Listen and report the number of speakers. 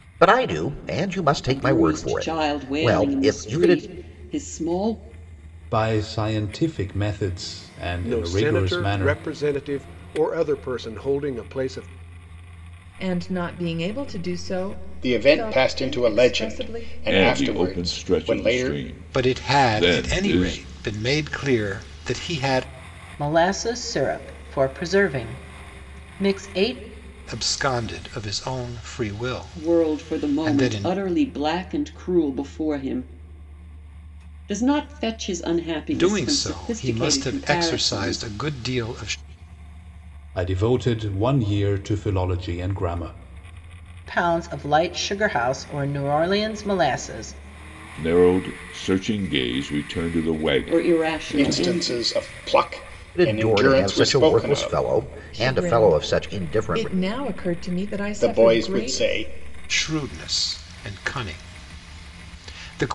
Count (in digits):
9